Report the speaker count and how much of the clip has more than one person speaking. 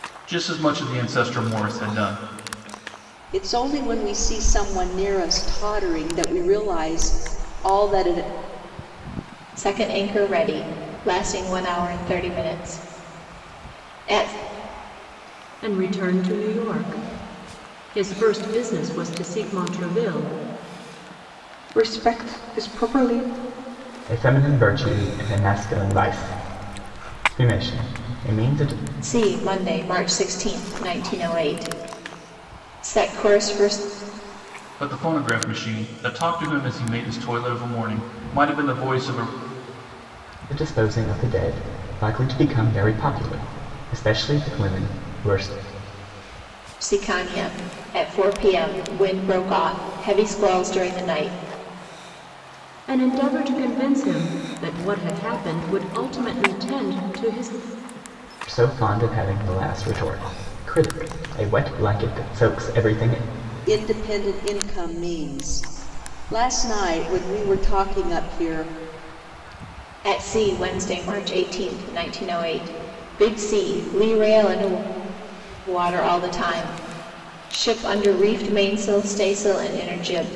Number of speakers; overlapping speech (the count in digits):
6, no overlap